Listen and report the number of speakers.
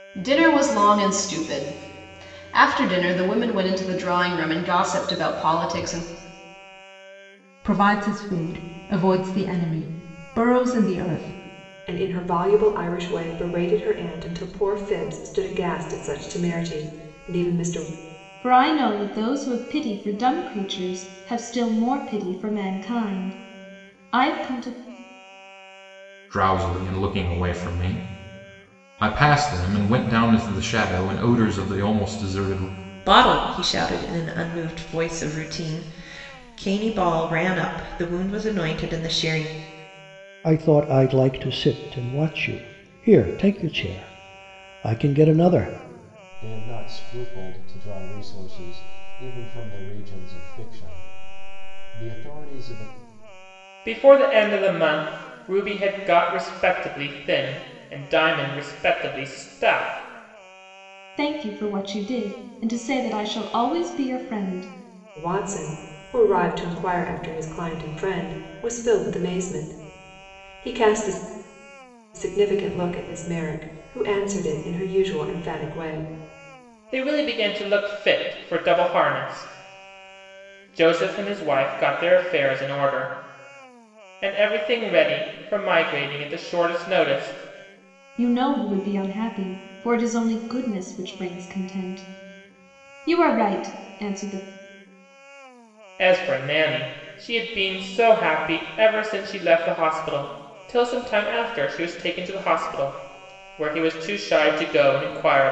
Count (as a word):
nine